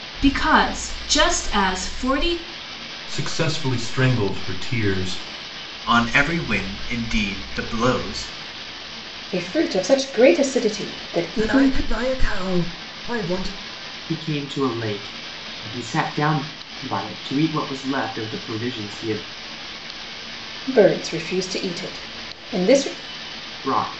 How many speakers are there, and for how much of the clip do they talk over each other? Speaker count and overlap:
6, about 1%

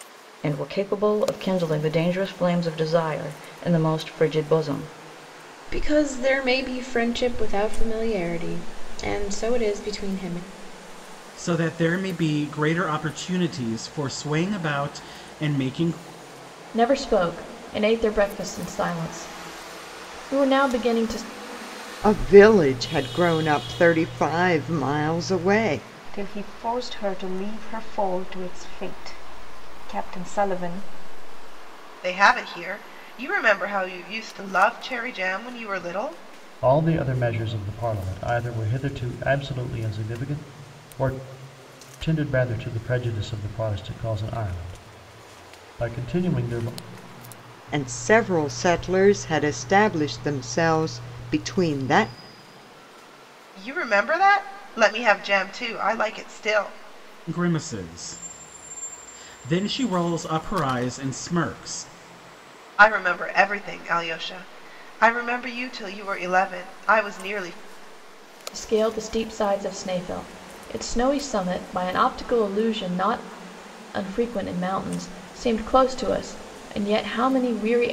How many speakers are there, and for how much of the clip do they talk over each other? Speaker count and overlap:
8, no overlap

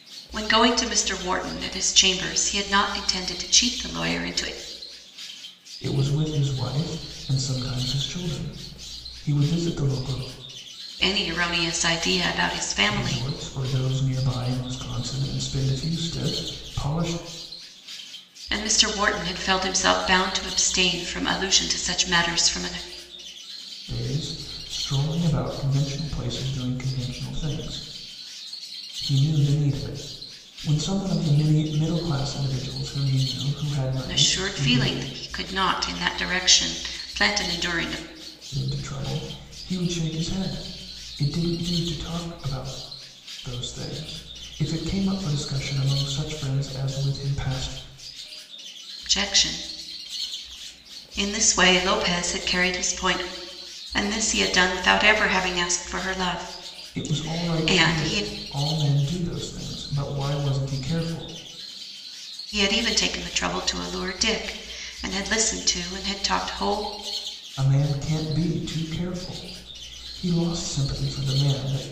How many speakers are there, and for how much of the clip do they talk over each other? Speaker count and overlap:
2, about 4%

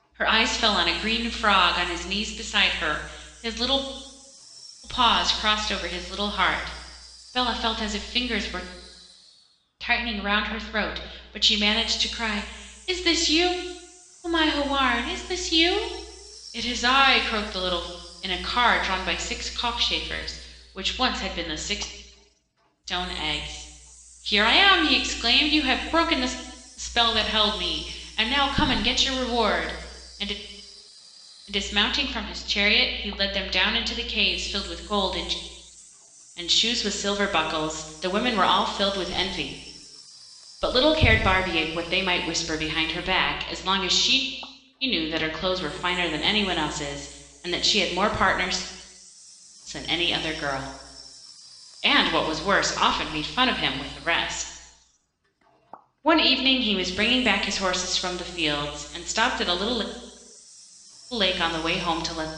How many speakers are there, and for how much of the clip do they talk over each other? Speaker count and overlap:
1, no overlap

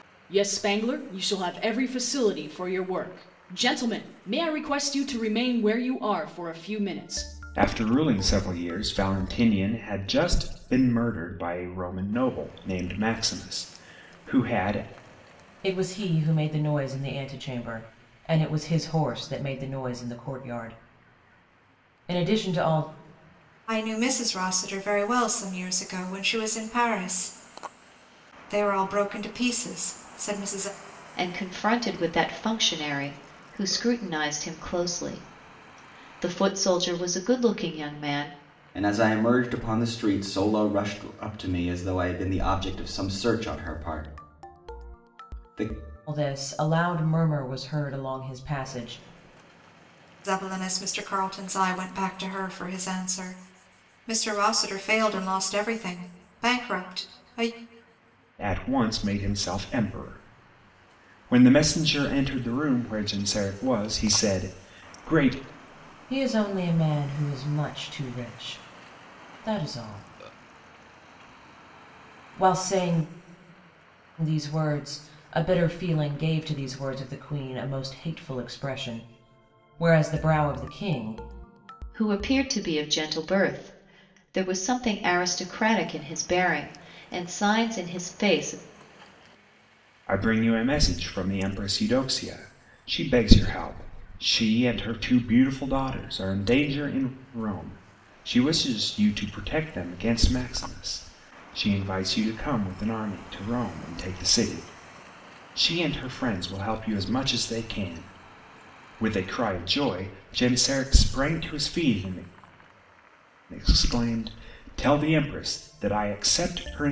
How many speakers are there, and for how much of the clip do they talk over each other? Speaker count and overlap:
6, no overlap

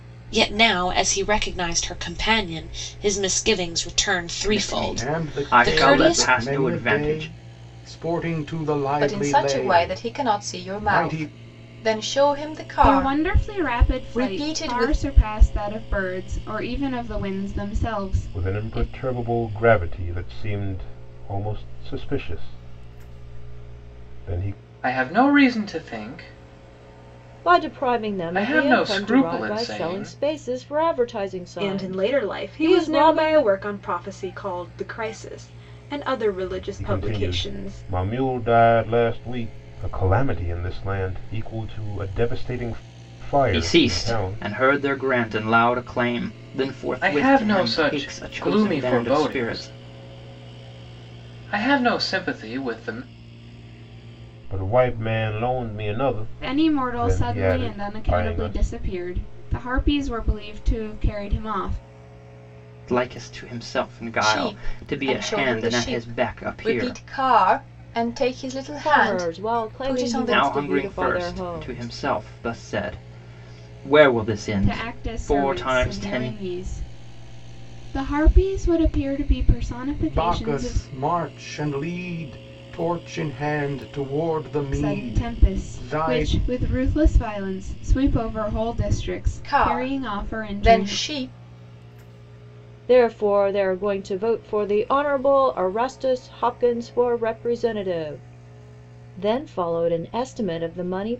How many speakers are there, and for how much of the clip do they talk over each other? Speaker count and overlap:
9, about 31%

